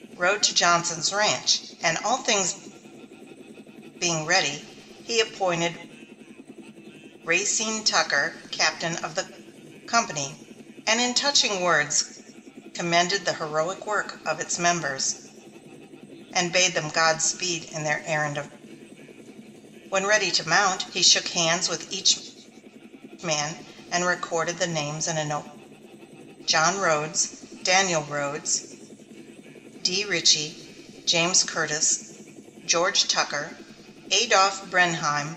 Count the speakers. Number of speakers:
one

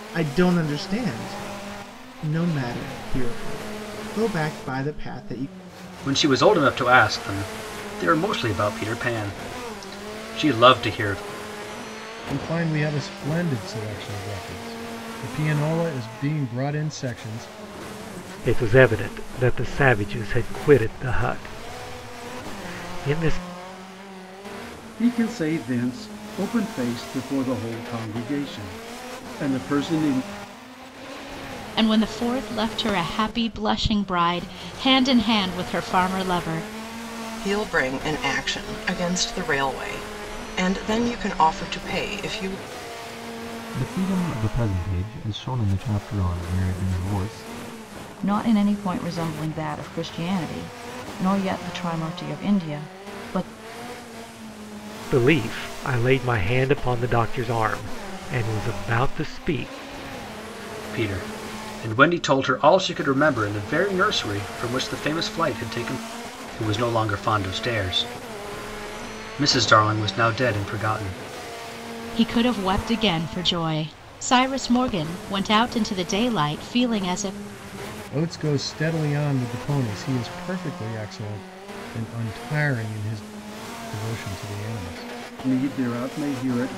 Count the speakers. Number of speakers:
nine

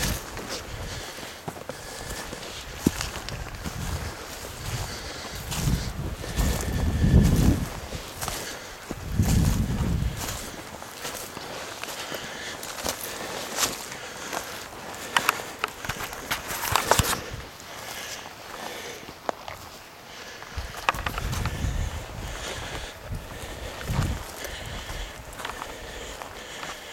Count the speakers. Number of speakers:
zero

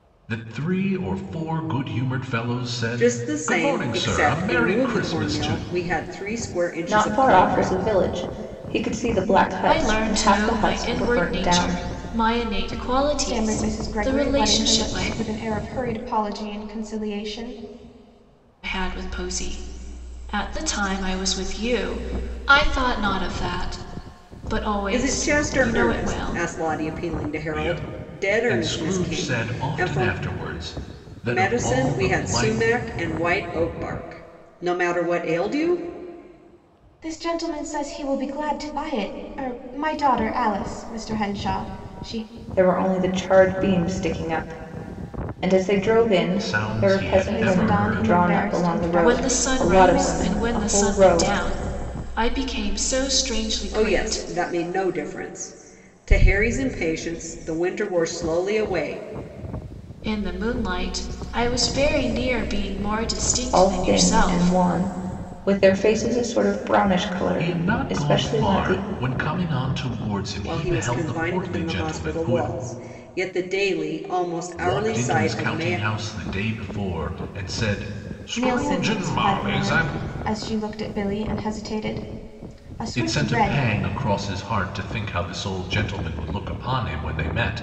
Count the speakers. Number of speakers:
five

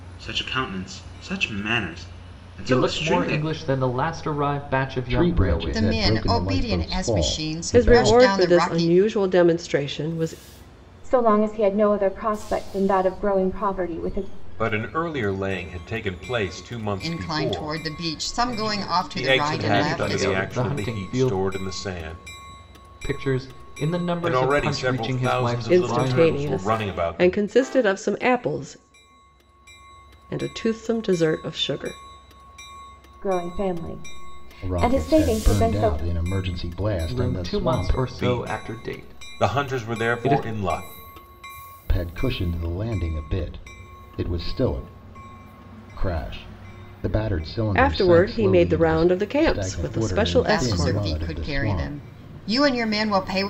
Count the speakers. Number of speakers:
seven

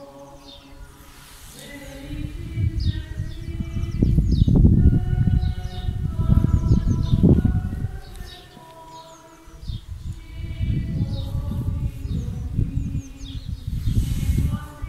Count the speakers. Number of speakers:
zero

